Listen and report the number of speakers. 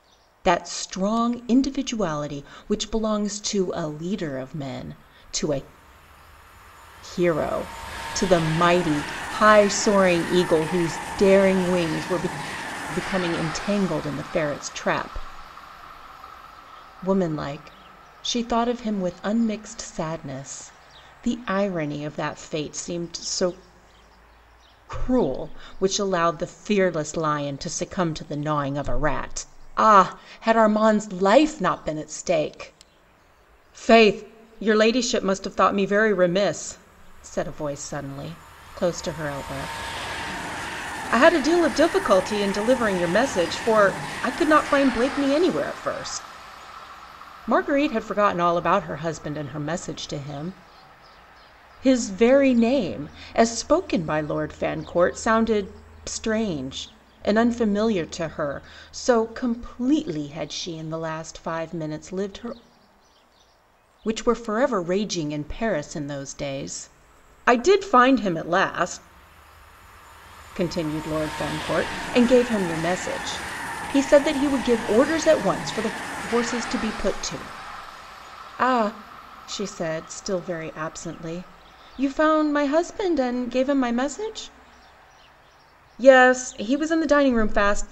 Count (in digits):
1